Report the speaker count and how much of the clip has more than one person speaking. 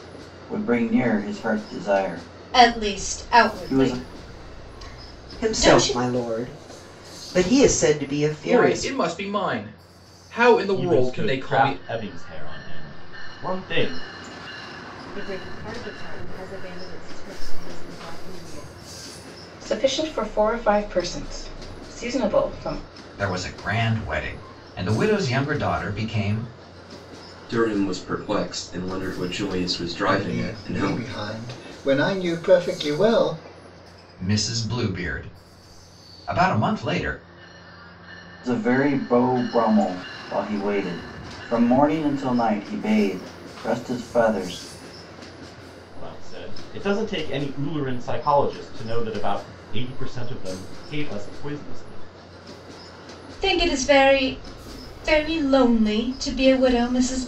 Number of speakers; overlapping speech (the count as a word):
ten, about 8%